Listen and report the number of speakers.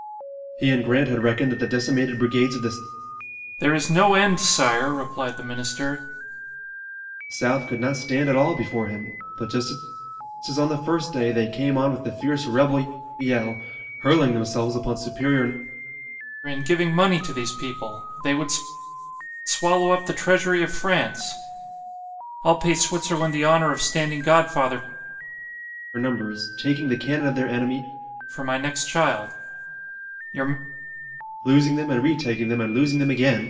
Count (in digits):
2